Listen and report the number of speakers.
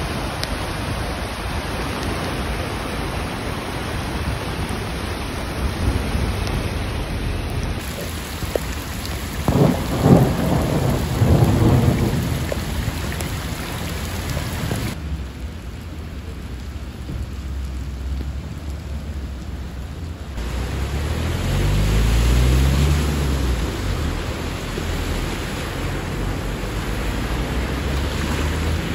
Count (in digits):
0